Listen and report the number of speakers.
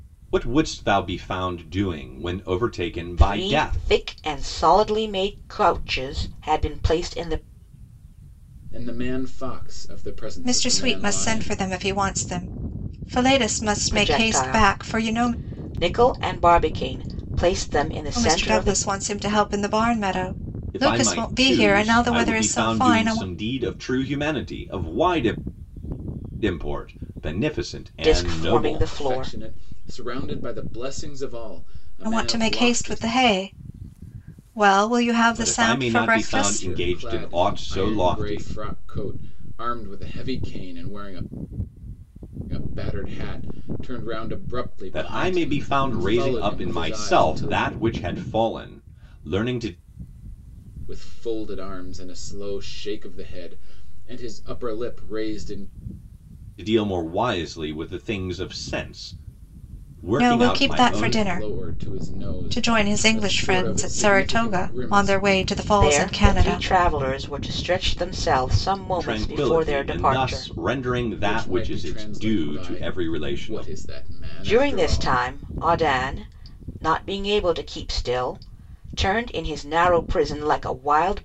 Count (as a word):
four